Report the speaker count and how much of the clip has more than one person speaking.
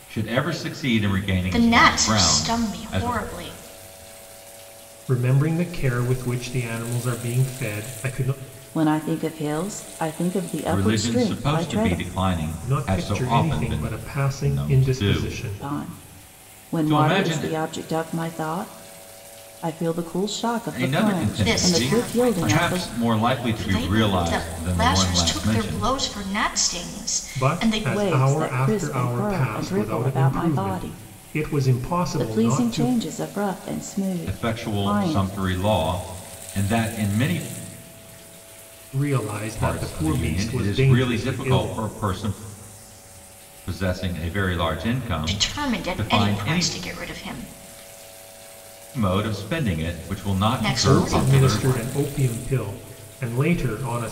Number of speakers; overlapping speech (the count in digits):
4, about 43%